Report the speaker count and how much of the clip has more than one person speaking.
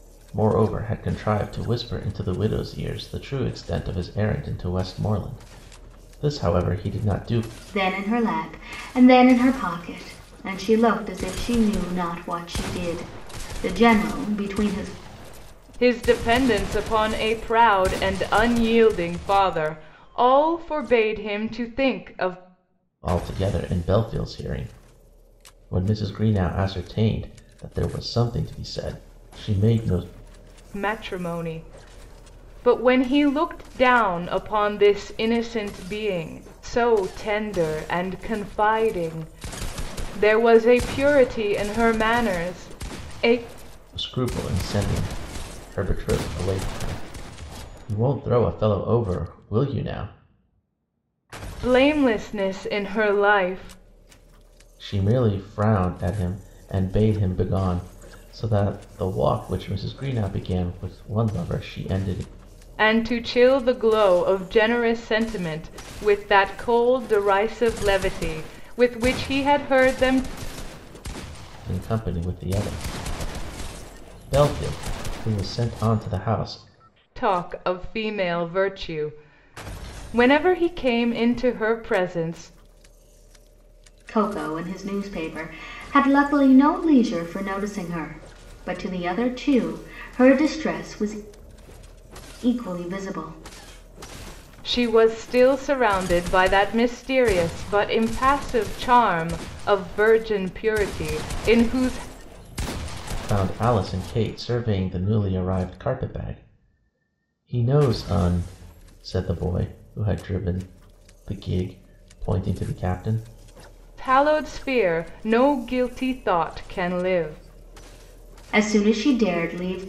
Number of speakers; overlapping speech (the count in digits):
3, no overlap